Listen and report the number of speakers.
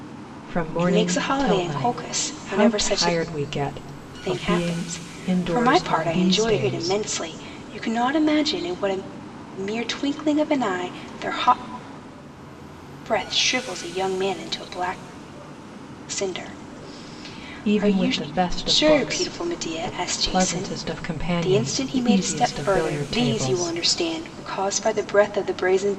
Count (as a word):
two